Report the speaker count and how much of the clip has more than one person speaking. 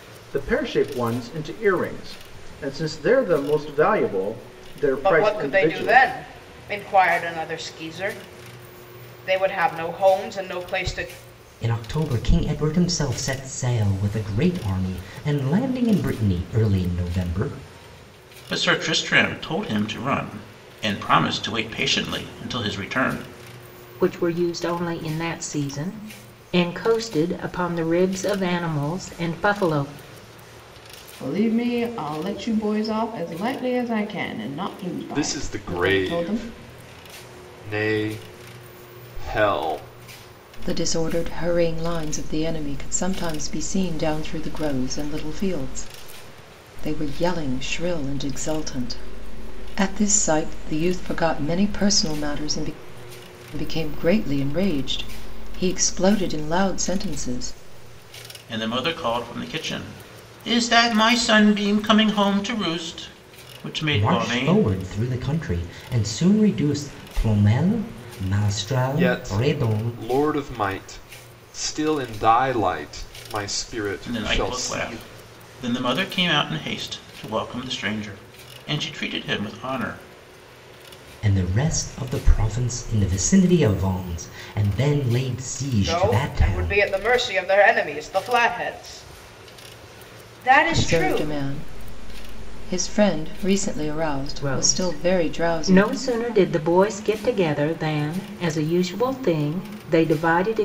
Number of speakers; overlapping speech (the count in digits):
8, about 8%